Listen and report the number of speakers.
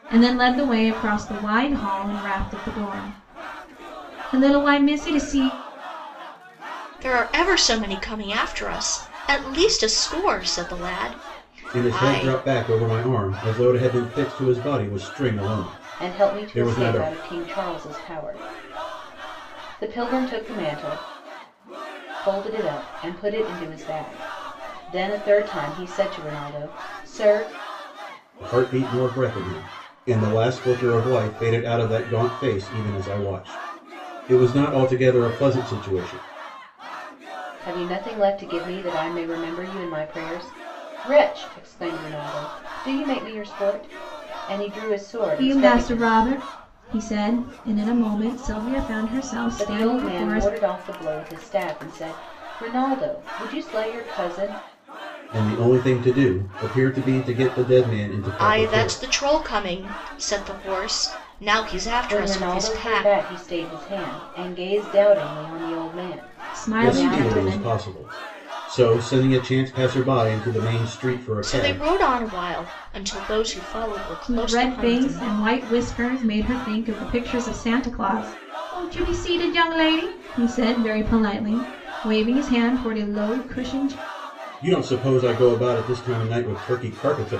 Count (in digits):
4